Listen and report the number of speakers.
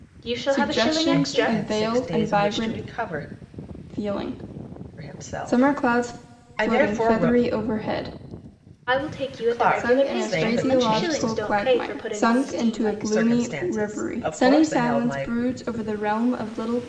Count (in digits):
3